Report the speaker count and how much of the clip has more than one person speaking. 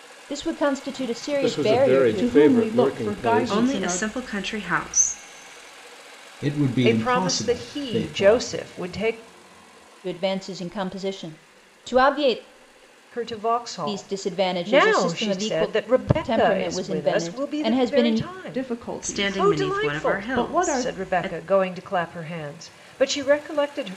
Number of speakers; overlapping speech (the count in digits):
6, about 48%